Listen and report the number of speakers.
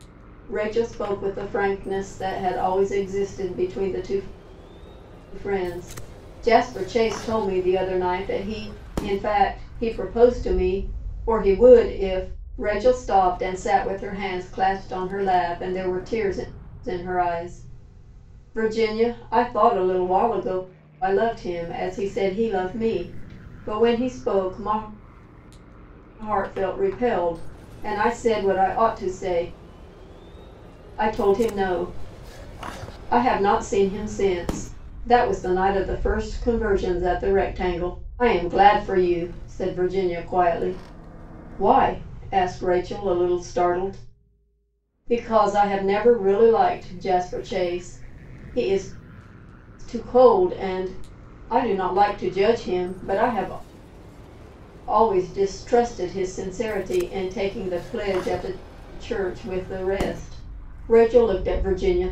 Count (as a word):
one